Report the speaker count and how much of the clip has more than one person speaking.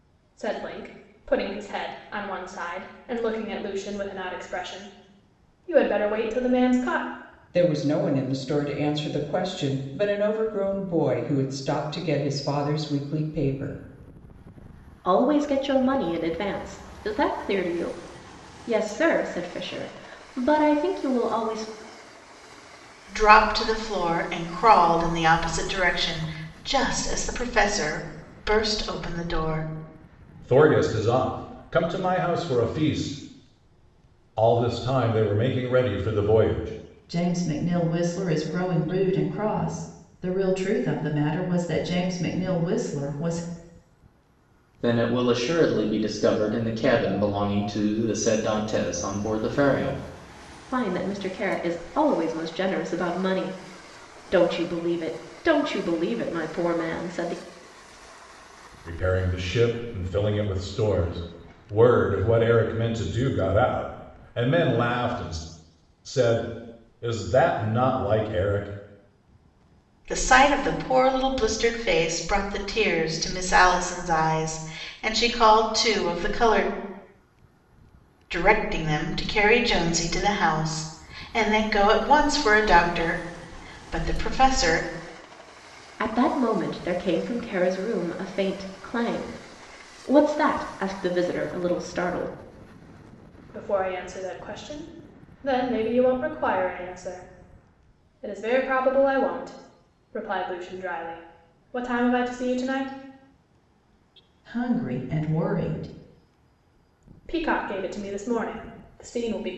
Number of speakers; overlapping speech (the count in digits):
7, no overlap